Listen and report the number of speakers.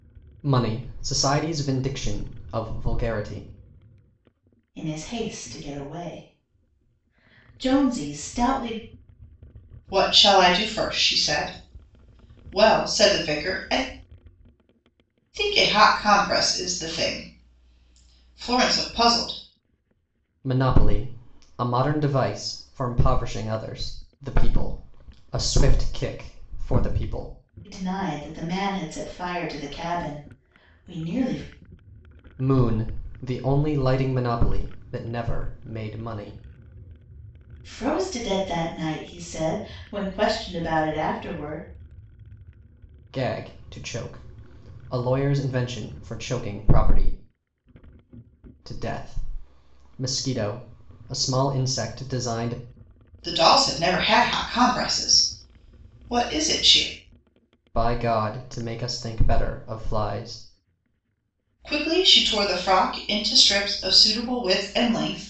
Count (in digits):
3